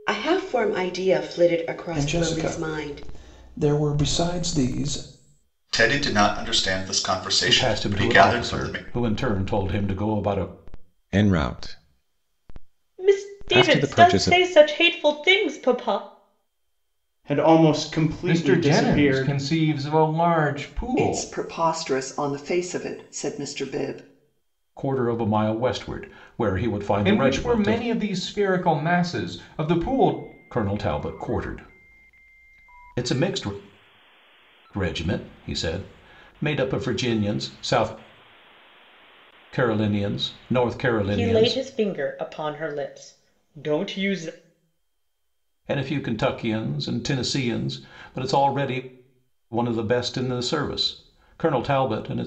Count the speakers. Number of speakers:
9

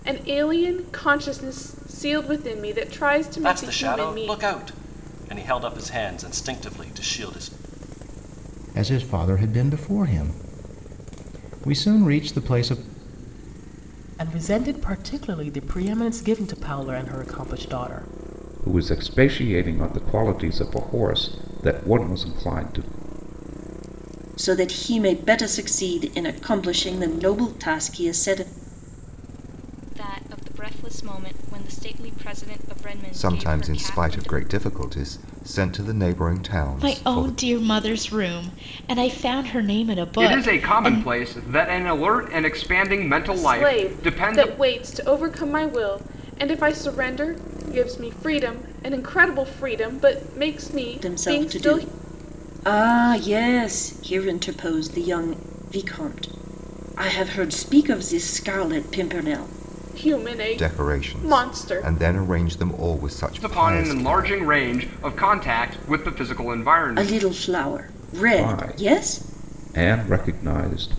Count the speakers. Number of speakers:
10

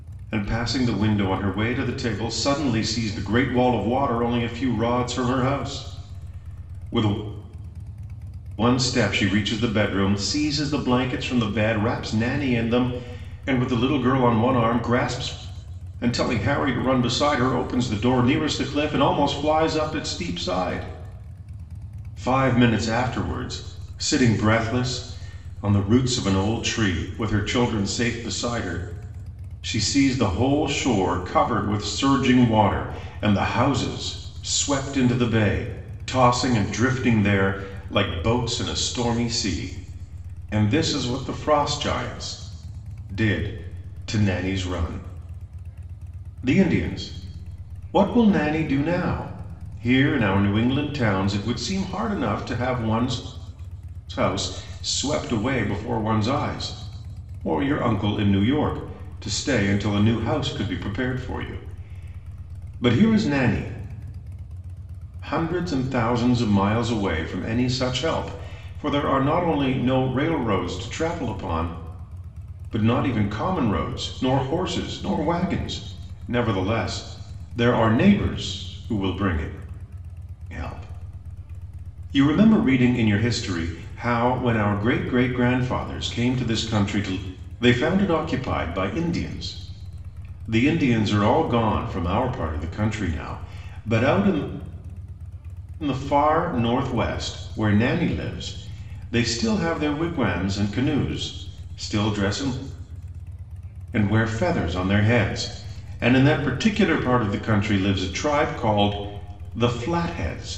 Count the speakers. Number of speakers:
1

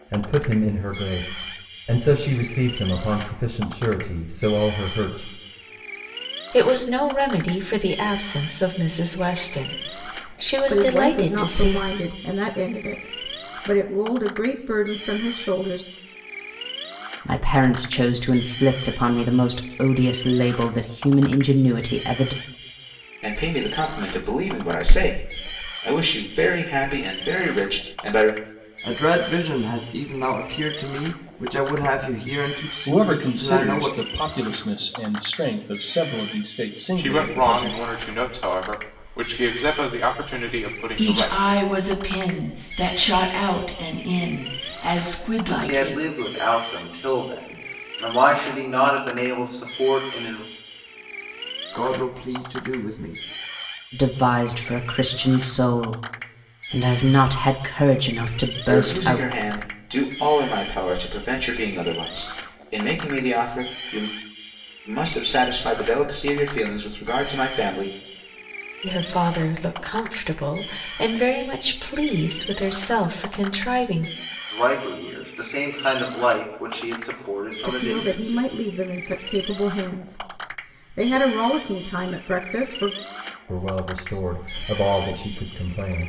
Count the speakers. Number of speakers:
10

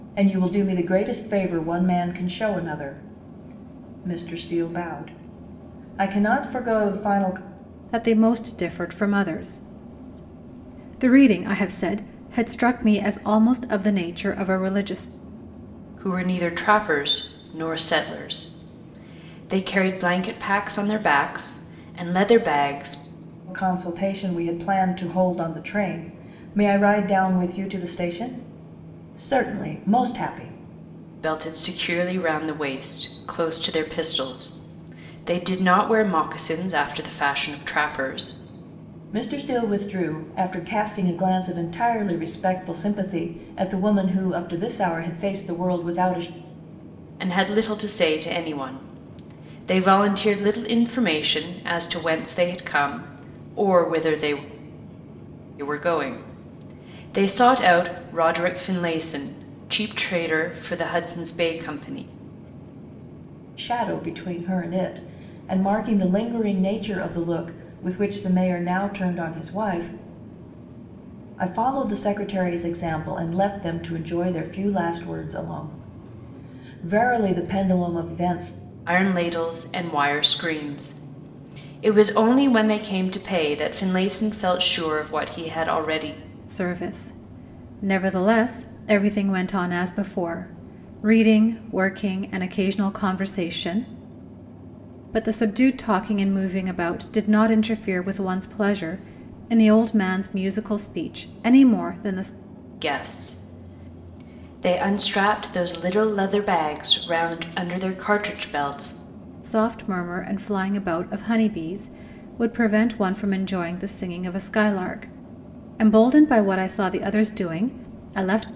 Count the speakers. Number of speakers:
3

